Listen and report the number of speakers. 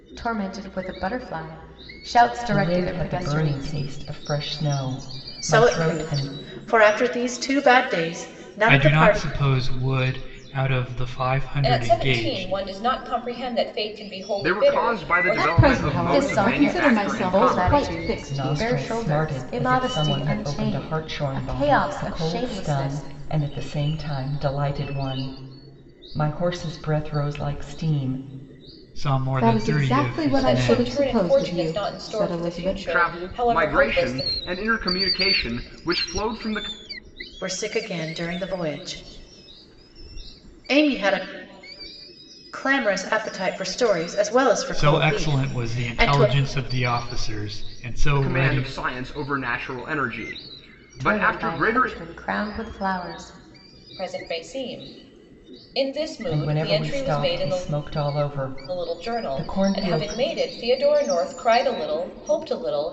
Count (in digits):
7